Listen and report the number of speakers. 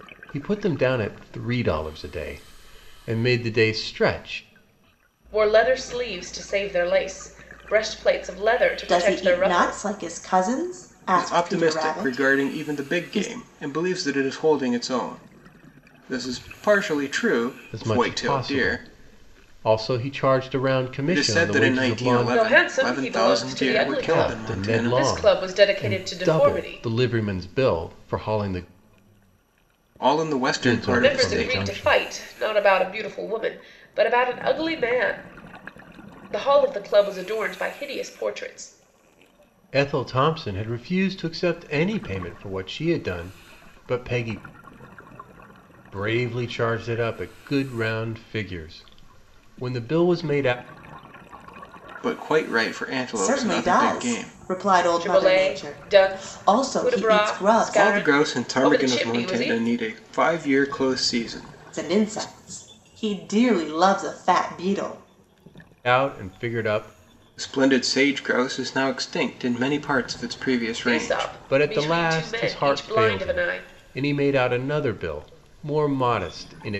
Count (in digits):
4